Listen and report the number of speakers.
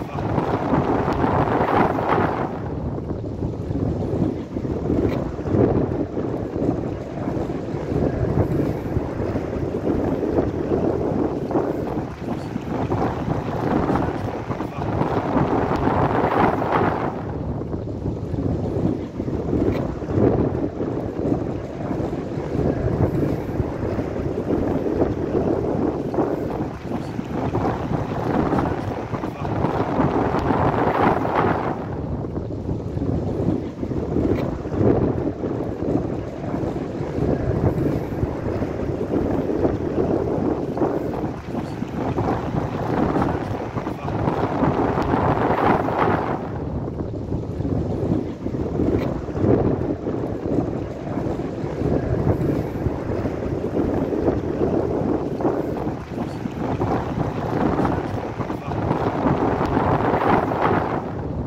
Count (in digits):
0